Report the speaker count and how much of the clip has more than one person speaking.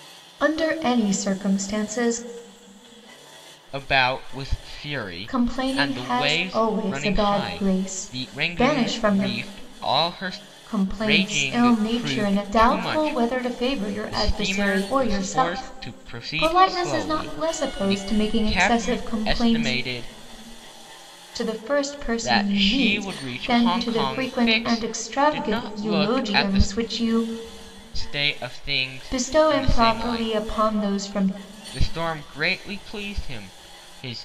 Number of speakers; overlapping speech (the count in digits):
2, about 52%